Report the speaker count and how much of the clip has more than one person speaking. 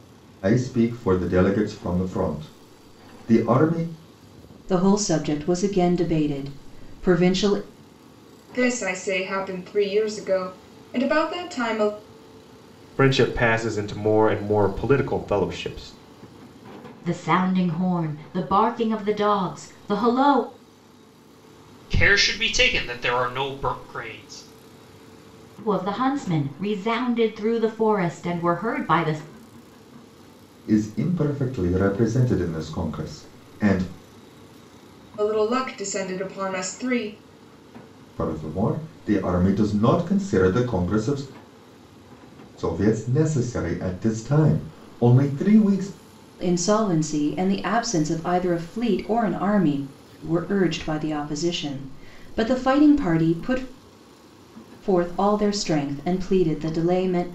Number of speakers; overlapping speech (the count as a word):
six, no overlap